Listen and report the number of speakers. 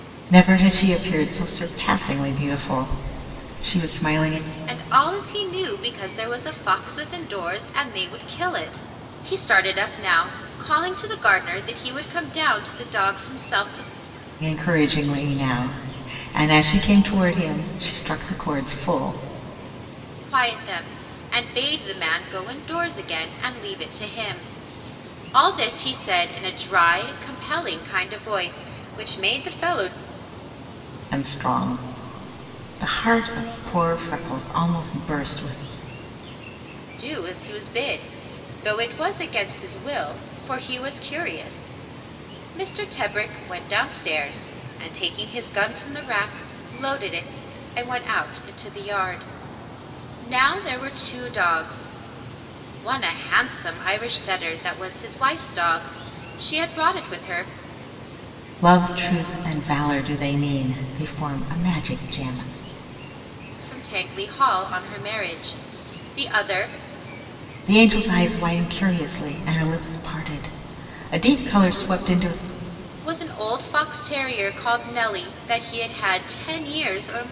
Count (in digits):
2